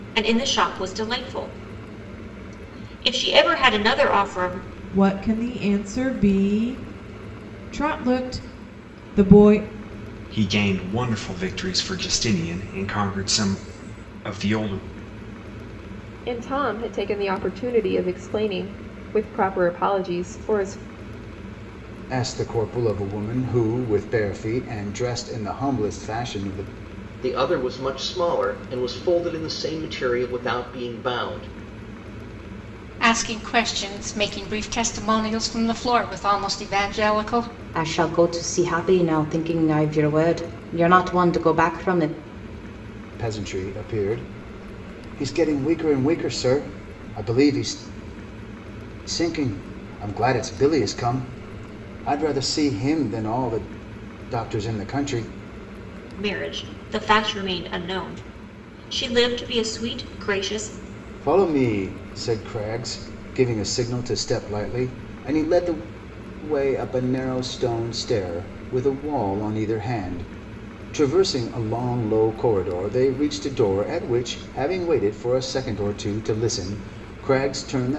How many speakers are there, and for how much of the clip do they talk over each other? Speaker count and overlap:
8, no overlap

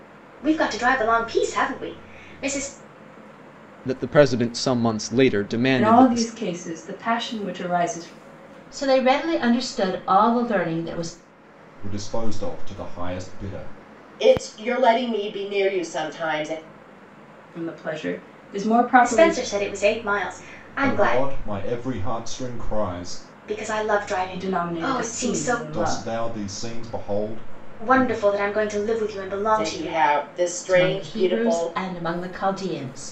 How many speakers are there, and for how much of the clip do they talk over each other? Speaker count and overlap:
6, about 15%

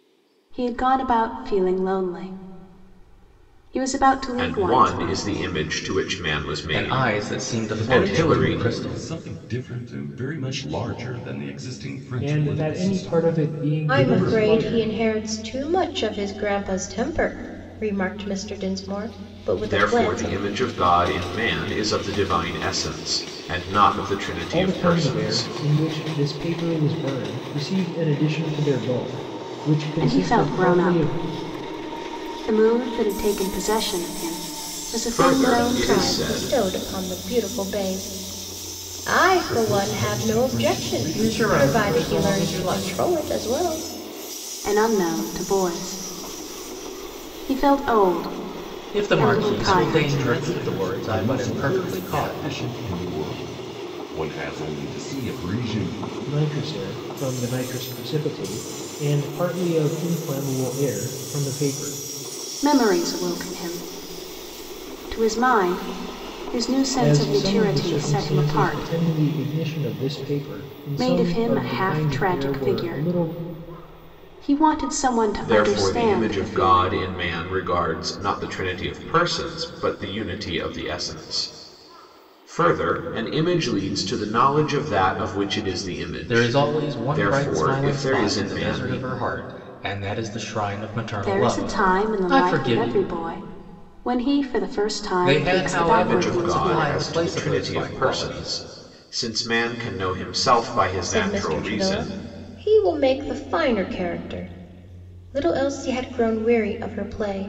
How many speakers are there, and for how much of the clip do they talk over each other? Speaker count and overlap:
6, about 30%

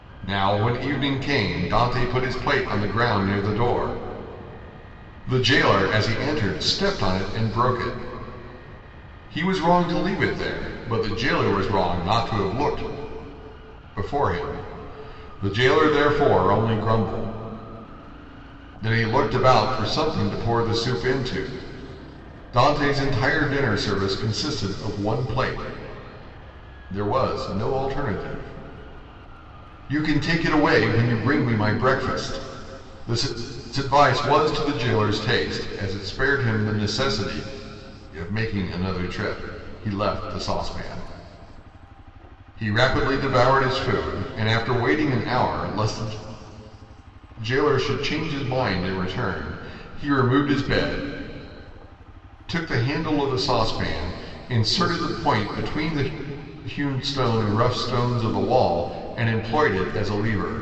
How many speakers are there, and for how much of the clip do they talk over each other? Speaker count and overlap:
1, no overlap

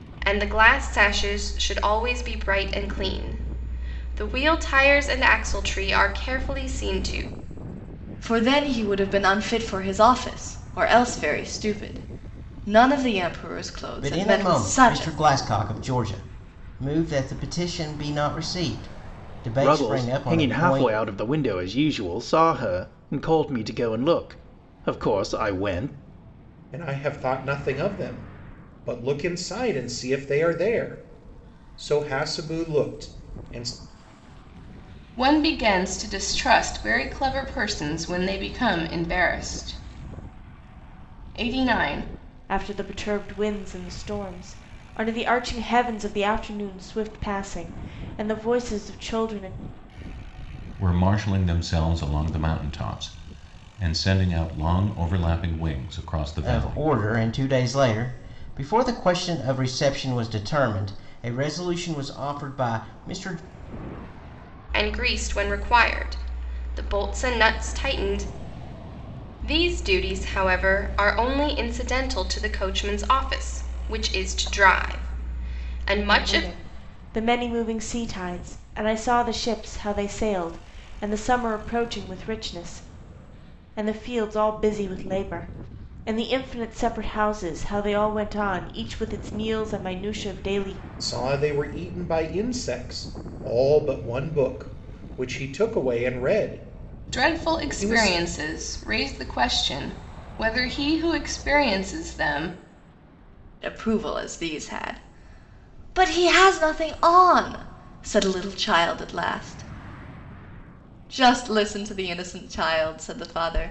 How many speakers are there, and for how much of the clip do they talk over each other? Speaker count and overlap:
8, about 4%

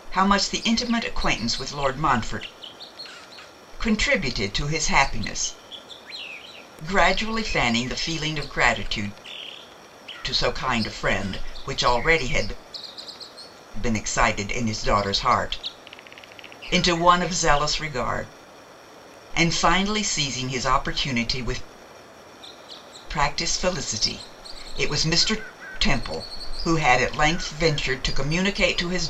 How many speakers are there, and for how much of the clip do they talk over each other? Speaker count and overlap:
1, no overlap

